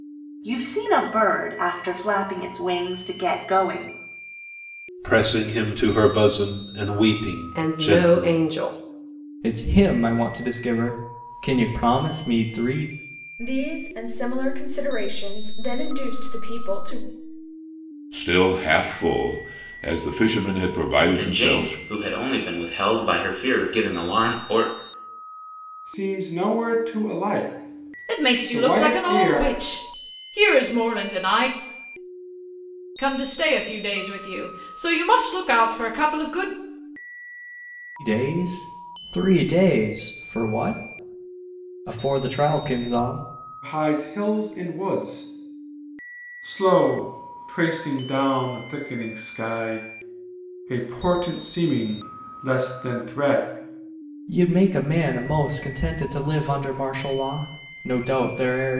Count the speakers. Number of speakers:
9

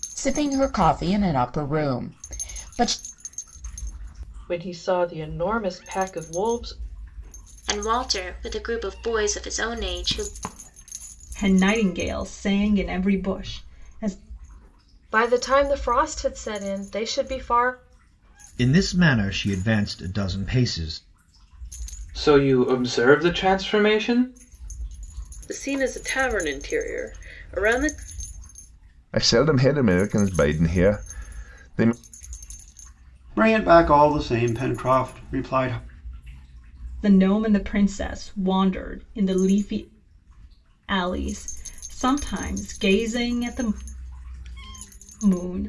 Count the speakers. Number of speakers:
10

